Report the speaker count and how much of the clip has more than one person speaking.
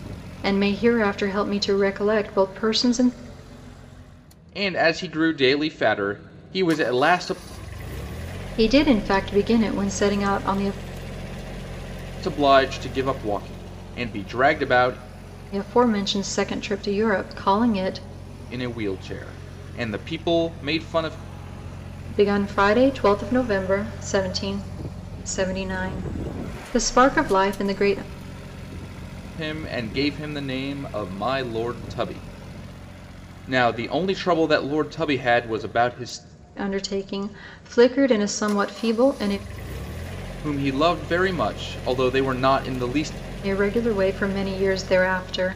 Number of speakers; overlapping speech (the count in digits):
2, no overlap